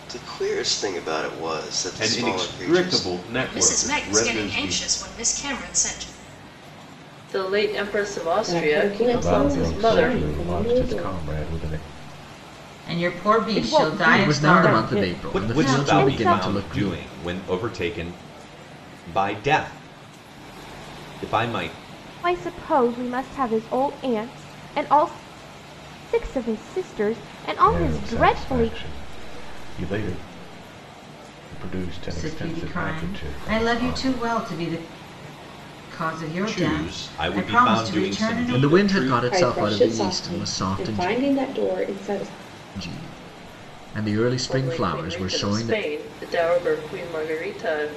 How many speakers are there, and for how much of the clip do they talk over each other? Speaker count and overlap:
10, about 38%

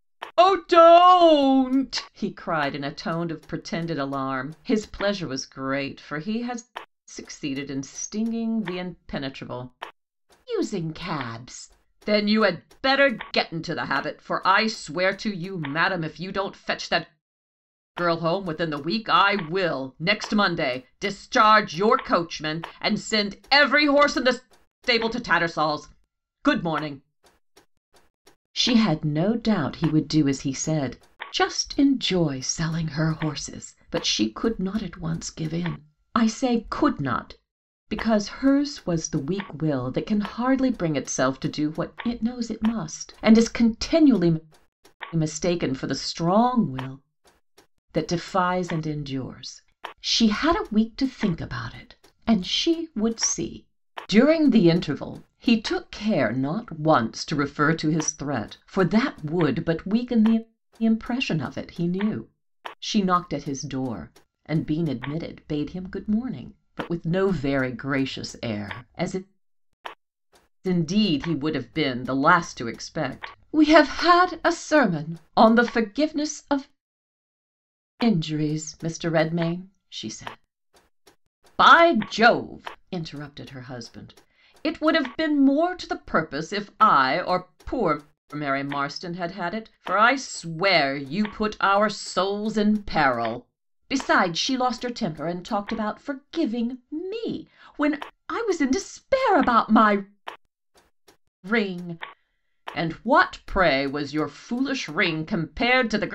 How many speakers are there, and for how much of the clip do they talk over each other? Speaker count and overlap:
1, no overlap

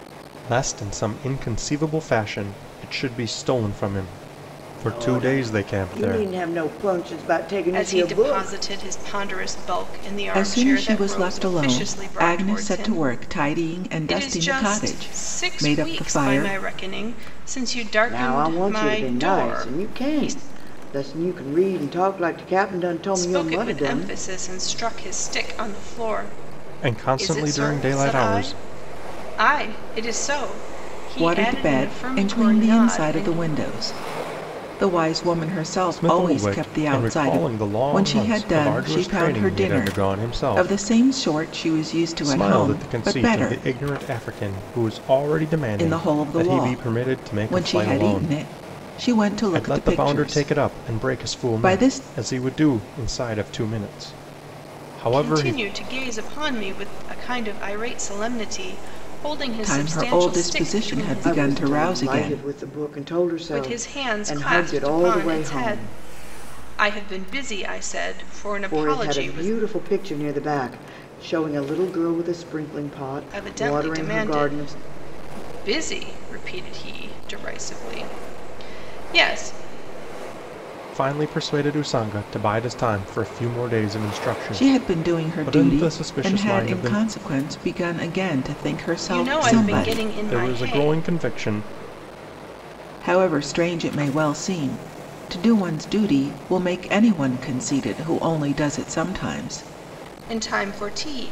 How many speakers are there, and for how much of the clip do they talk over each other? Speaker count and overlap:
4, about 38%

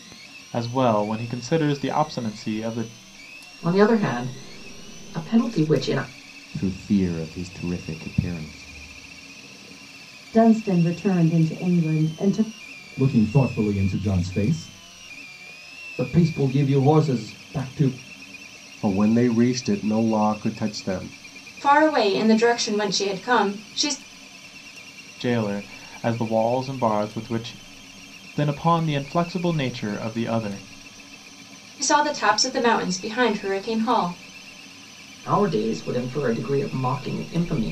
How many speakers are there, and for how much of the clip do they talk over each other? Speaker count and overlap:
8, no overlap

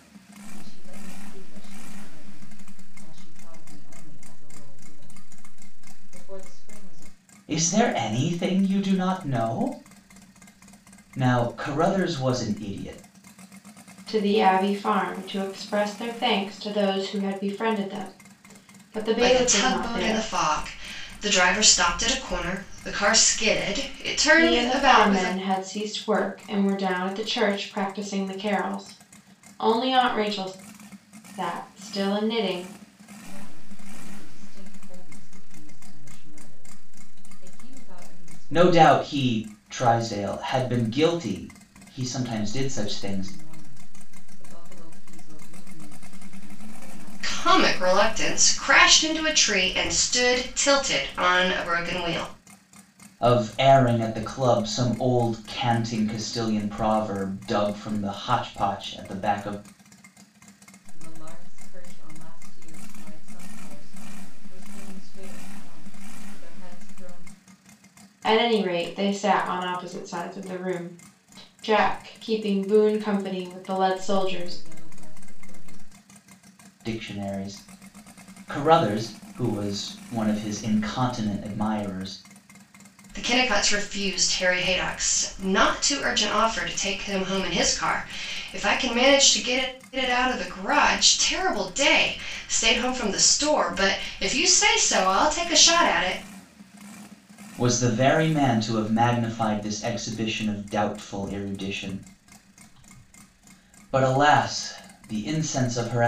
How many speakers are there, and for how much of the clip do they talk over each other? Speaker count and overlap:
4, about 5%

